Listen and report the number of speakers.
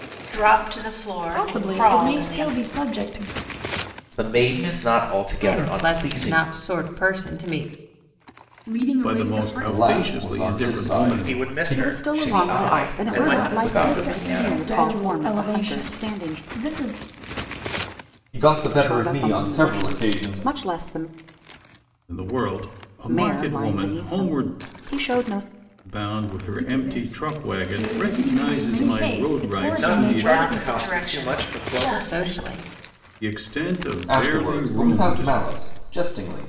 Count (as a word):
nine